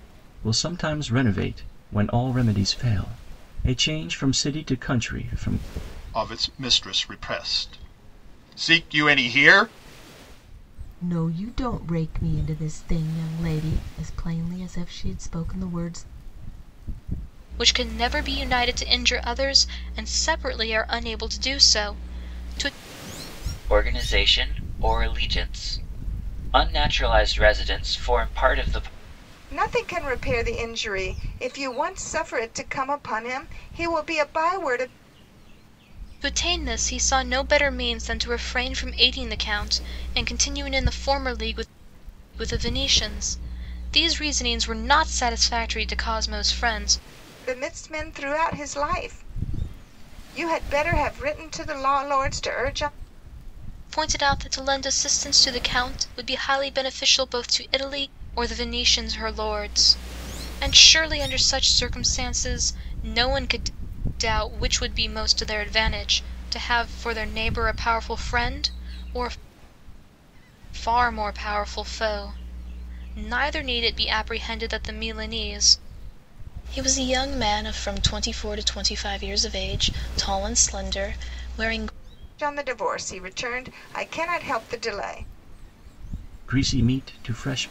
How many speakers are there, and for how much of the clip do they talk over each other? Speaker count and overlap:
six, no overlap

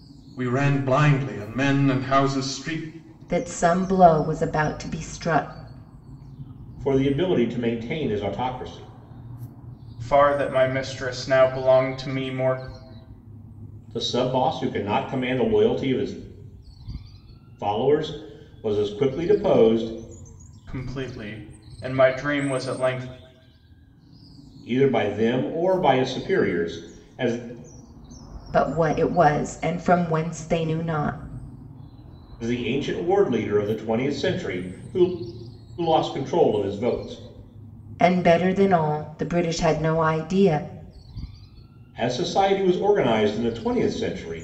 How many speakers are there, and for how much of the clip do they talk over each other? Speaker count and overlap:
four, no overlap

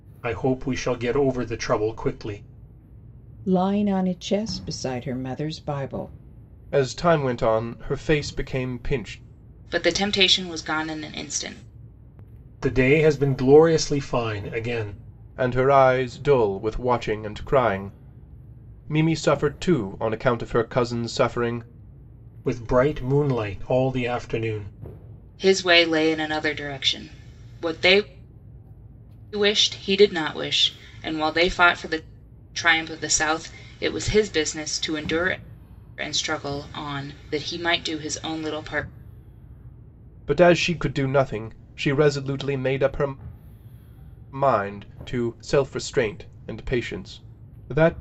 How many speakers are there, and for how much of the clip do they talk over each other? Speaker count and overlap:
four, no overlap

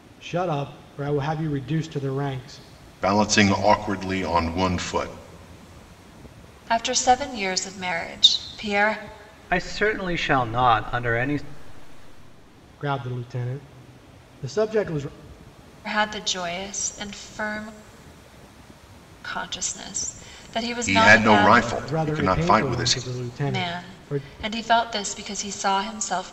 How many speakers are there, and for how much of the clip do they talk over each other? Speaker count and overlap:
four, about 11%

